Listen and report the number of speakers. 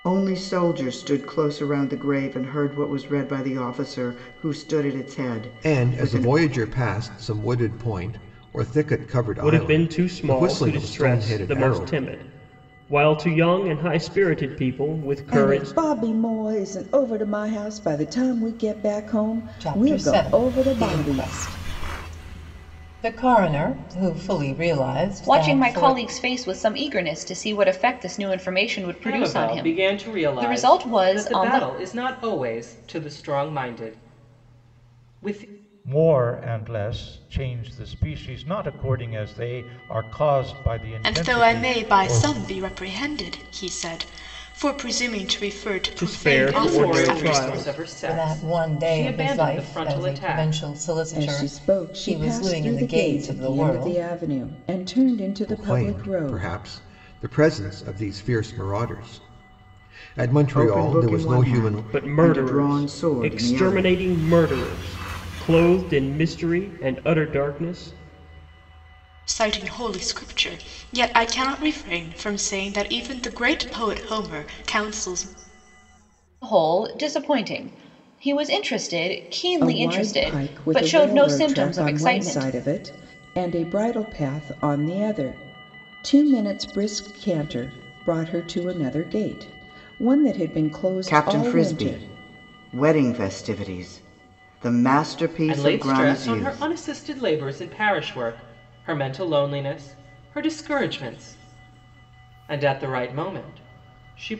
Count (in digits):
9